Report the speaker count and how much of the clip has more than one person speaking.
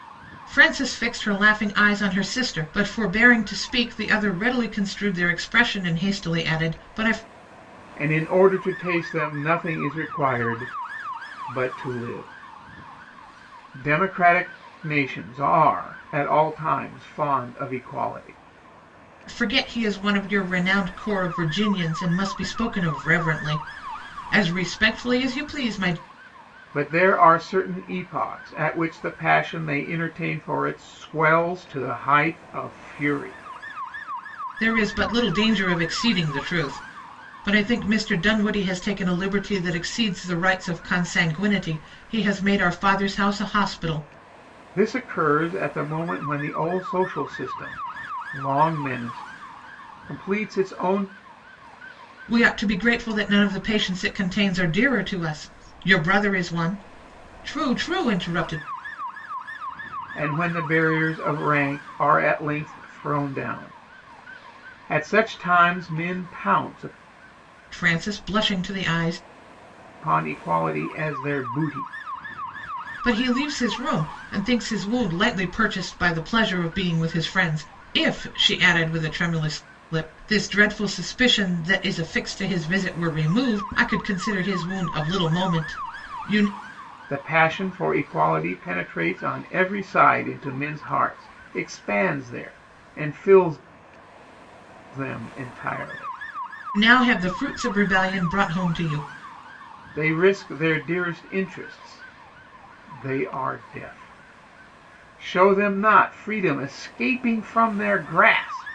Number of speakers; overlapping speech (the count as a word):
two, no overlap